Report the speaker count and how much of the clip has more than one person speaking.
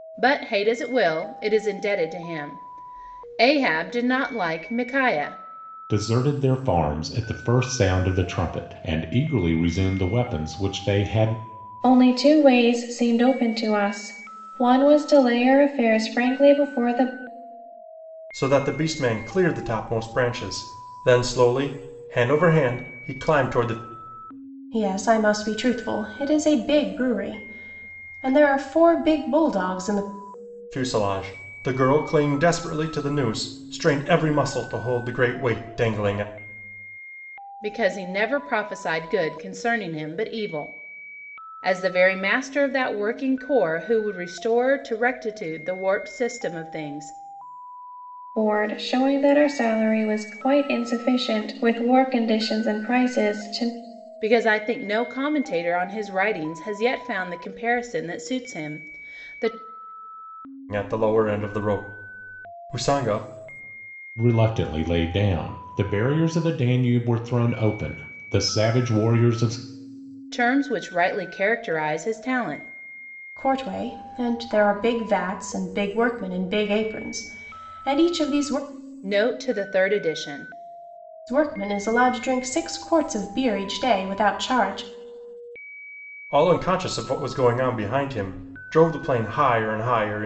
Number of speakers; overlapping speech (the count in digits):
5, no overlap